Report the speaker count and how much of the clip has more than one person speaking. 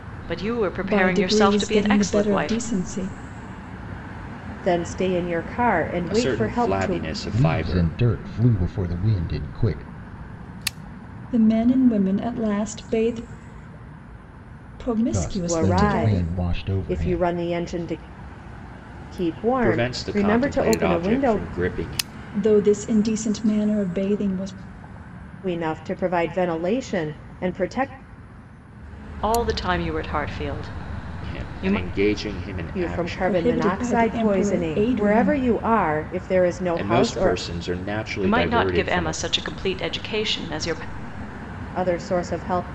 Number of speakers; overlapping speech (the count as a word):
five, about 29%